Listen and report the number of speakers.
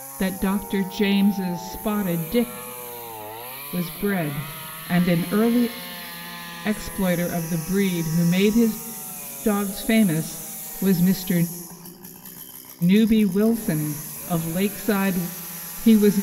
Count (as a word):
one